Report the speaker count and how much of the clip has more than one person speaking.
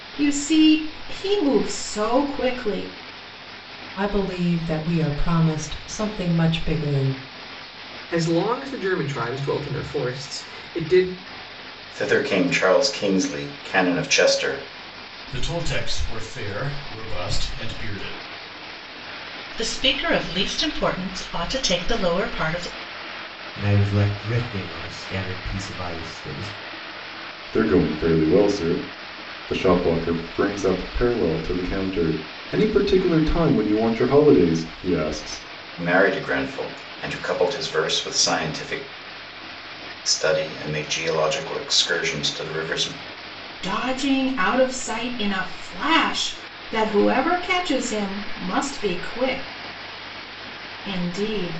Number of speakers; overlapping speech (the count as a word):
eight, no overlap